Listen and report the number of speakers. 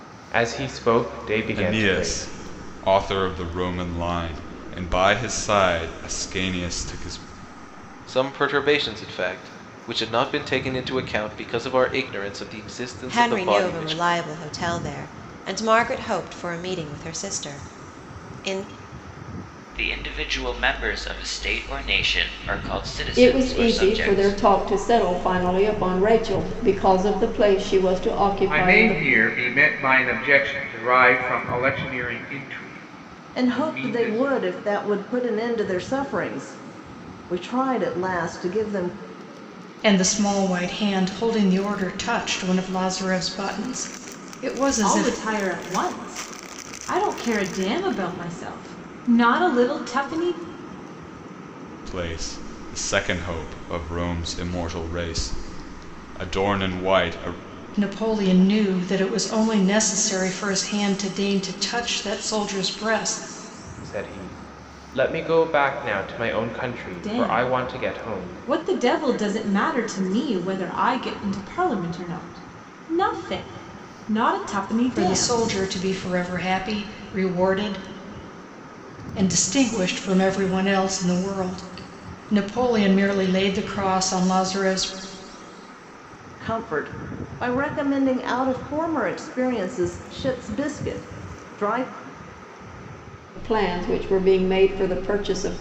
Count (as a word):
ten